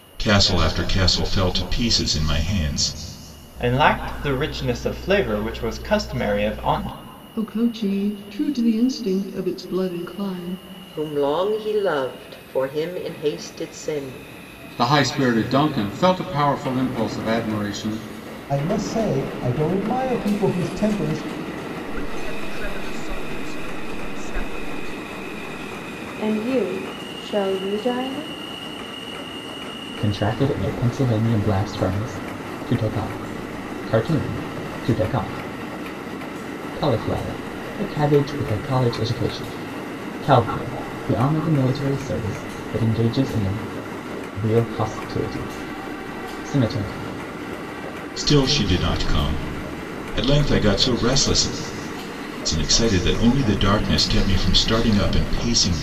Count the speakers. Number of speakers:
9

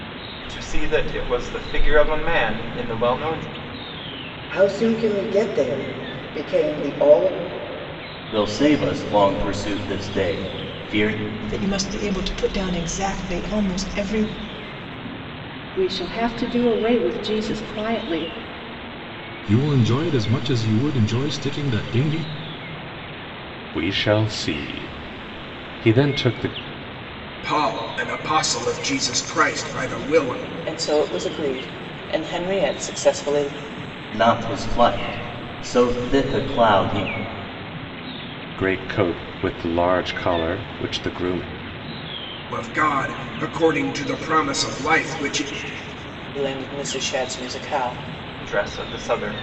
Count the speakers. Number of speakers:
9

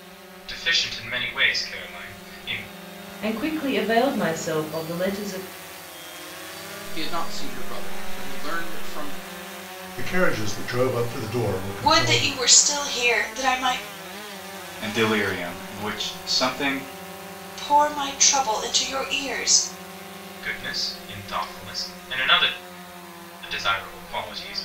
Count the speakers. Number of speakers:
6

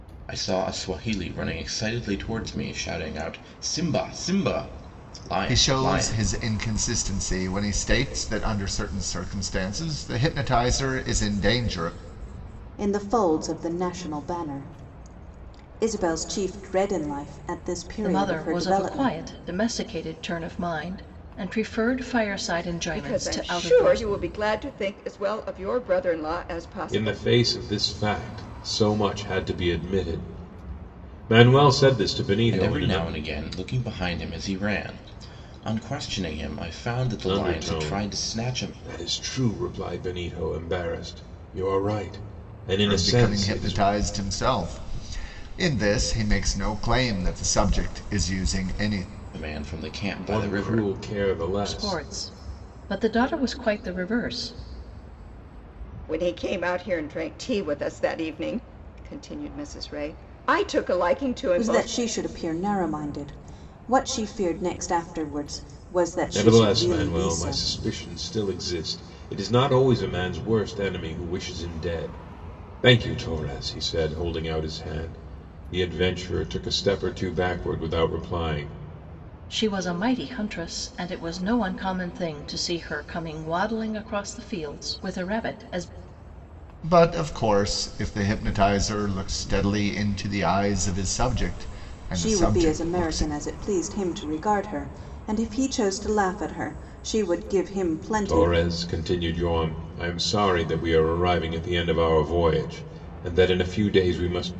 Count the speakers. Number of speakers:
6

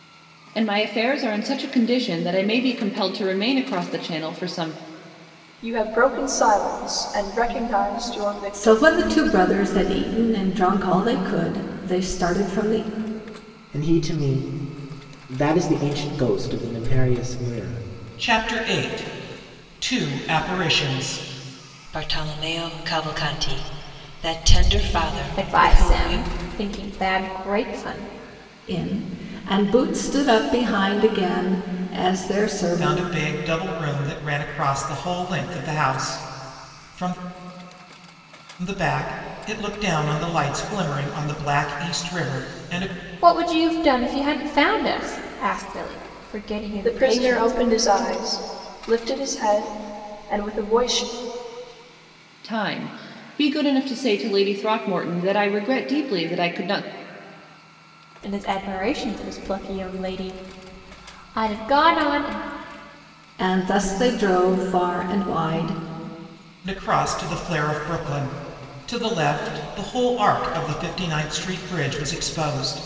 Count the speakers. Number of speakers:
7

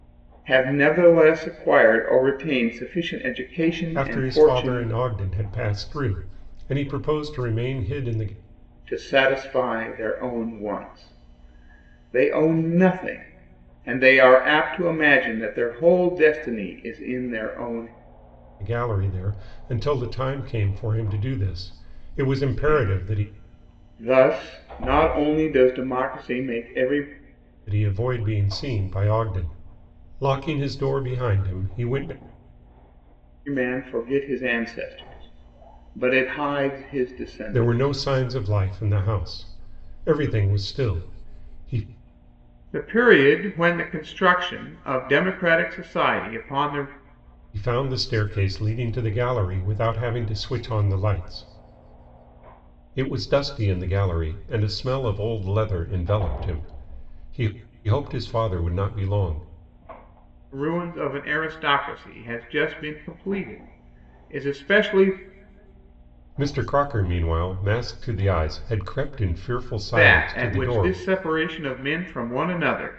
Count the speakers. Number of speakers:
2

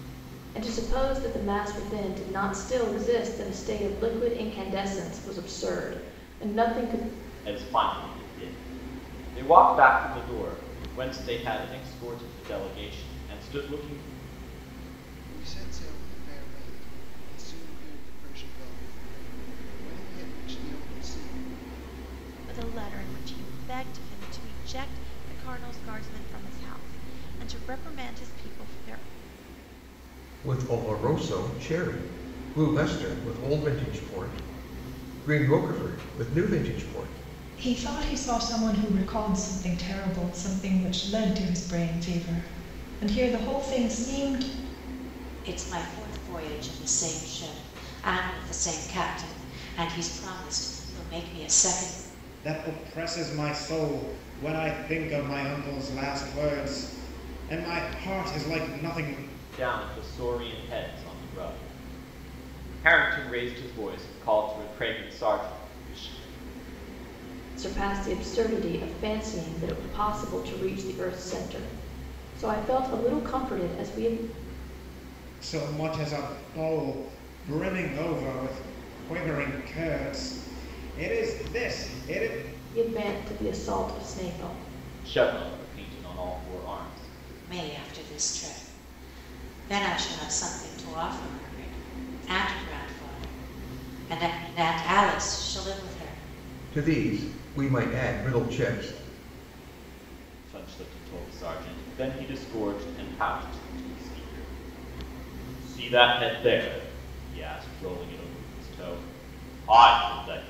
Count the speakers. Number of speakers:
8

